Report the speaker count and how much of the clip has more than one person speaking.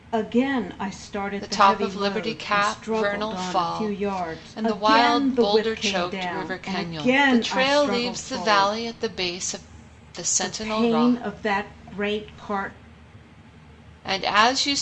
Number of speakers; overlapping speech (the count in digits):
2, about 57%